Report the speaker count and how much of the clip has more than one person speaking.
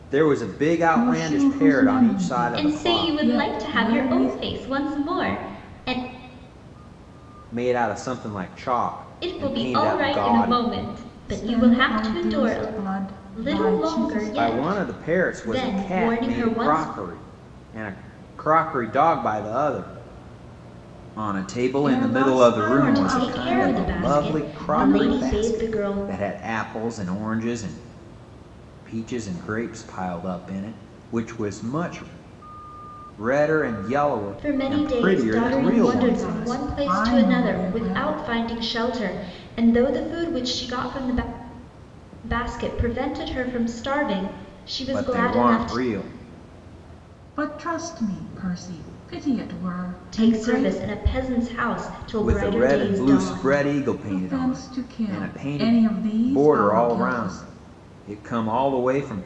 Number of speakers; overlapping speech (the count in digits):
3, about 41%